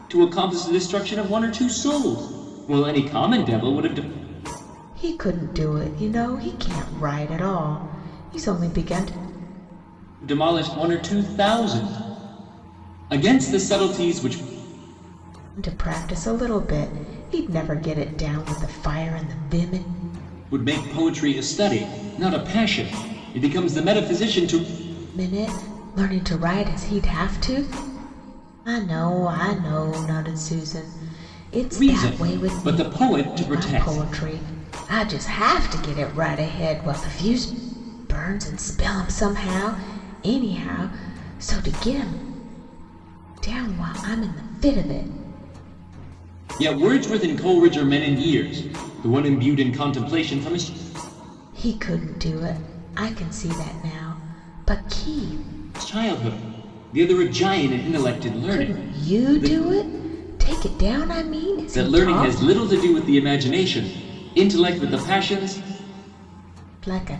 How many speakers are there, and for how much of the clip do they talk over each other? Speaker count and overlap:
2, about 6%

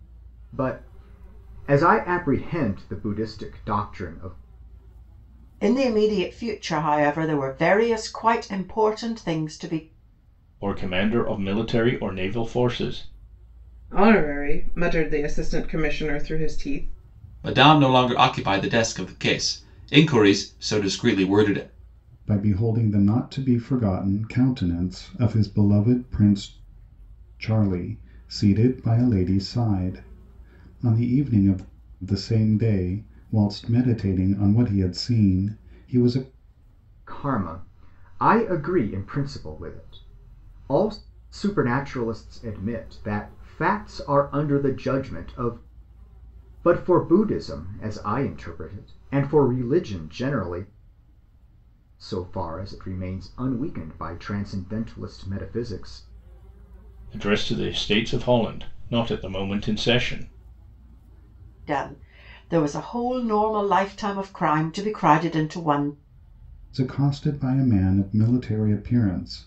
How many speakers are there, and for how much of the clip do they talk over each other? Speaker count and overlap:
6, no overlap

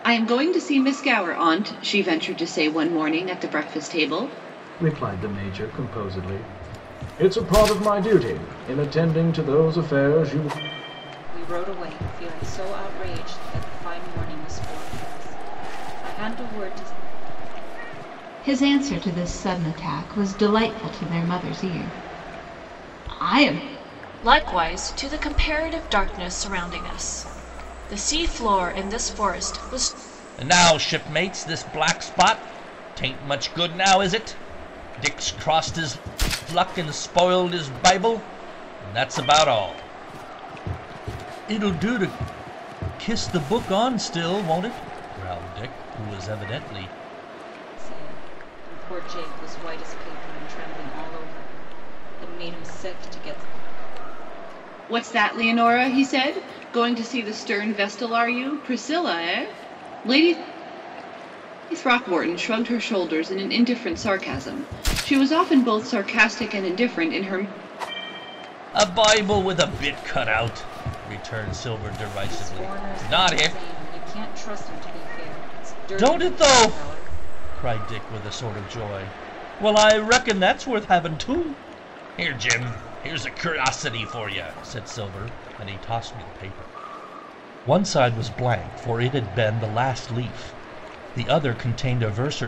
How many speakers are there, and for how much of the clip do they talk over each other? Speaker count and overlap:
6, about 3%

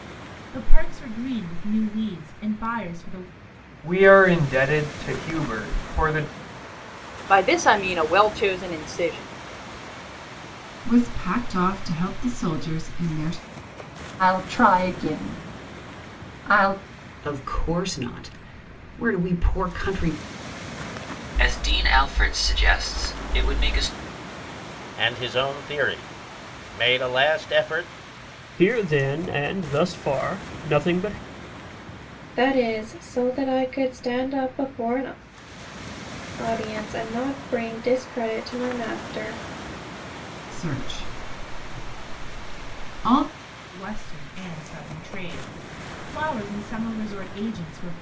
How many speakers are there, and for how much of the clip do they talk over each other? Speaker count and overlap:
10, no overlap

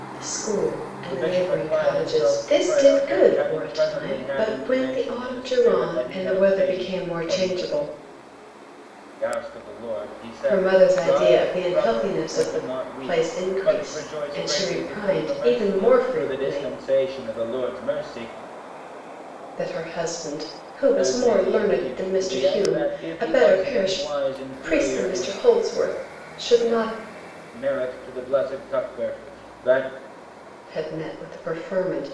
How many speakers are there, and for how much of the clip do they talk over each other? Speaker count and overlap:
2, about 50%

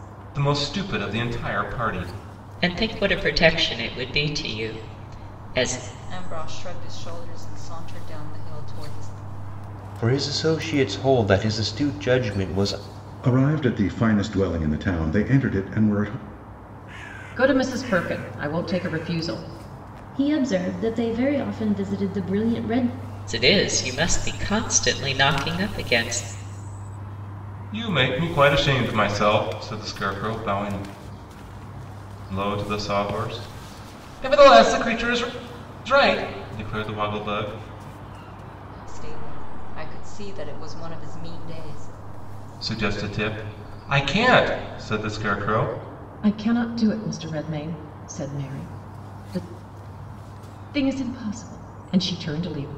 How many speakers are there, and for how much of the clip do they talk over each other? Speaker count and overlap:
7, no overlap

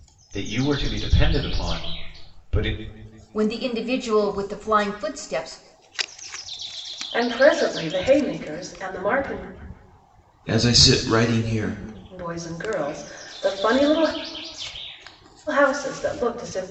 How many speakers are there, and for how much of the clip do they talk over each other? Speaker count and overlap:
4, no overlap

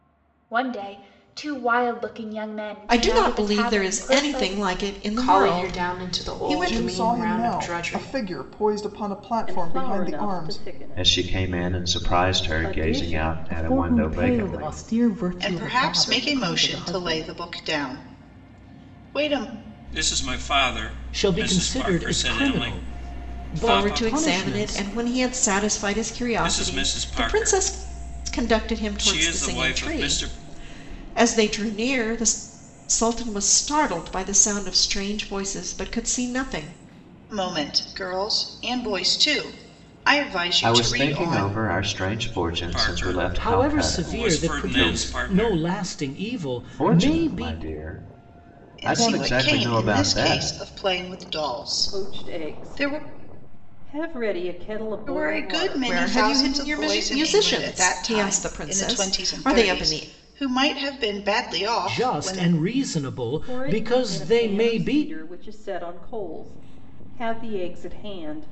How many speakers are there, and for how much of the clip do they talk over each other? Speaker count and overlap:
10, about 50%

